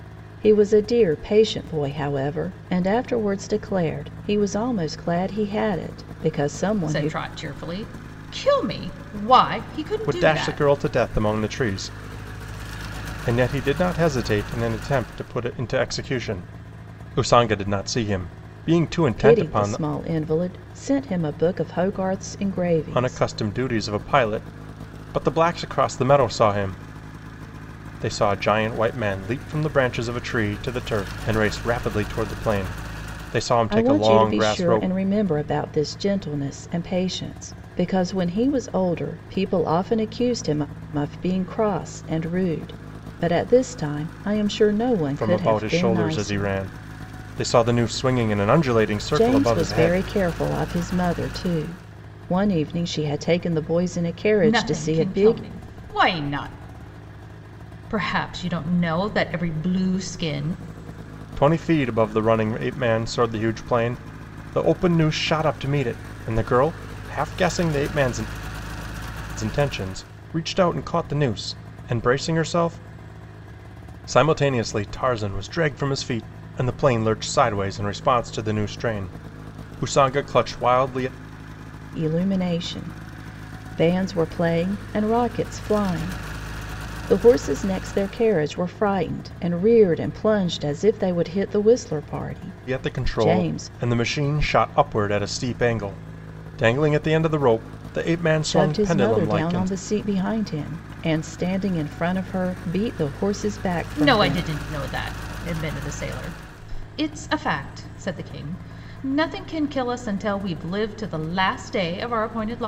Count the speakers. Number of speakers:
three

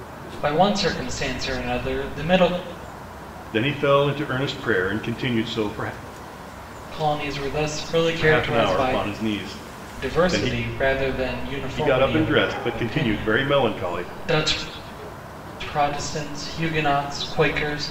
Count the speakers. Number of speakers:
two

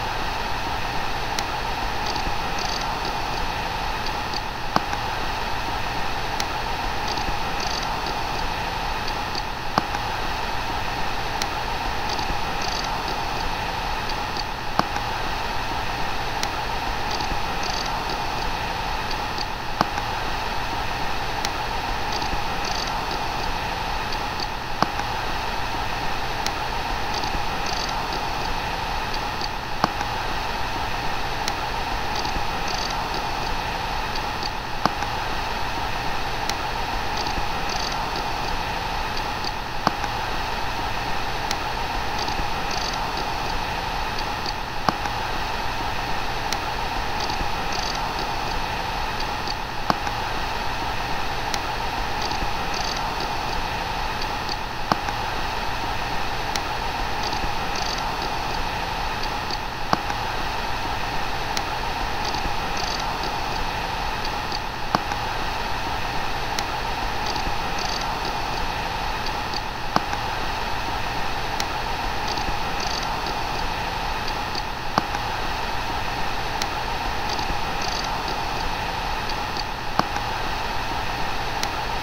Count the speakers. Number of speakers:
zero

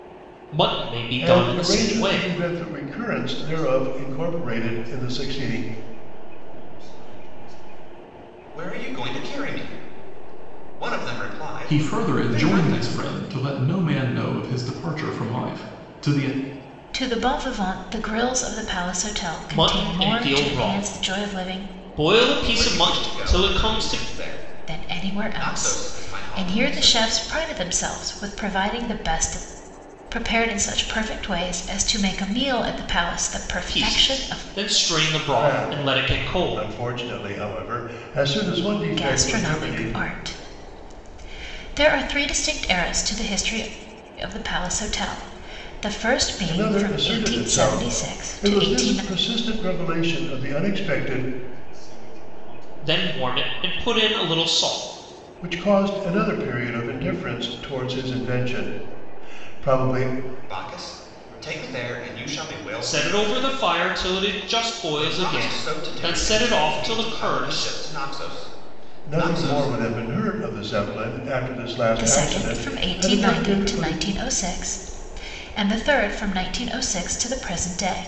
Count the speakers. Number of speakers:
six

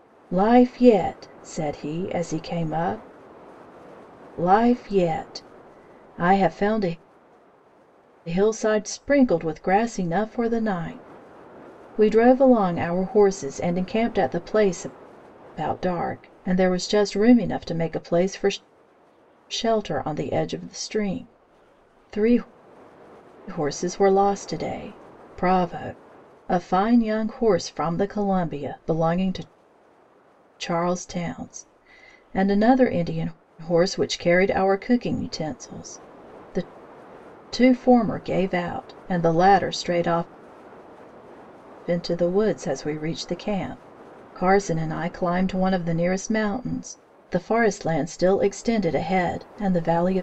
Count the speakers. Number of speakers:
one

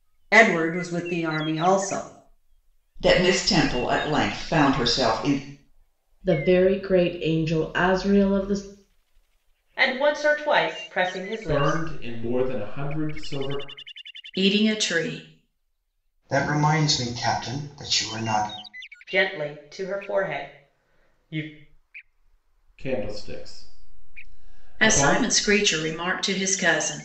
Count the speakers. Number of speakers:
seven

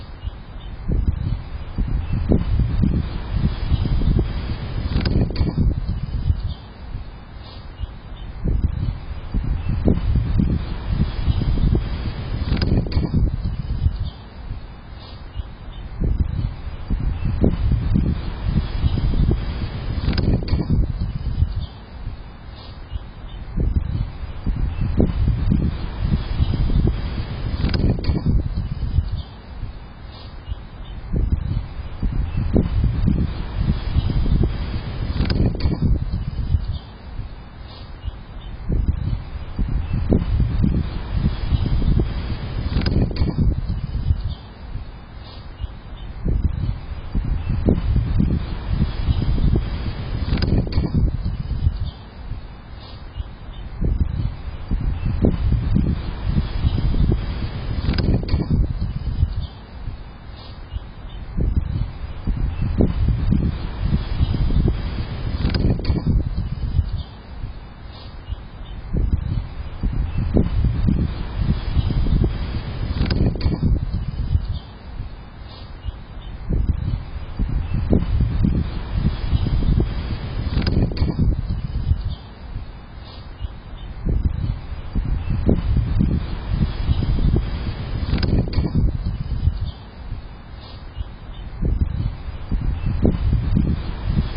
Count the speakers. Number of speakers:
zero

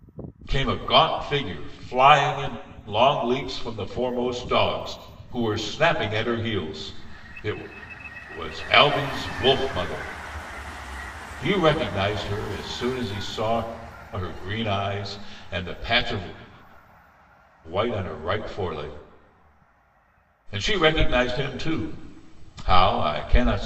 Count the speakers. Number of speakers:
one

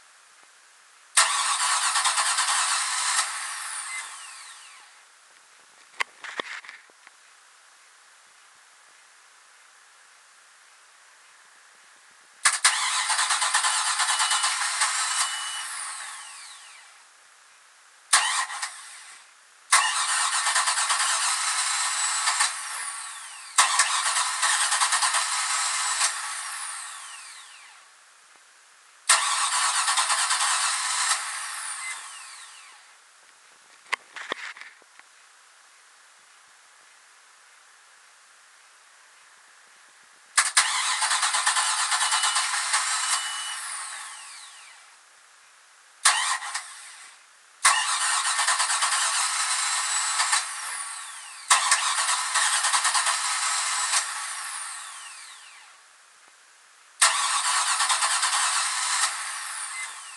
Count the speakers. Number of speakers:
zero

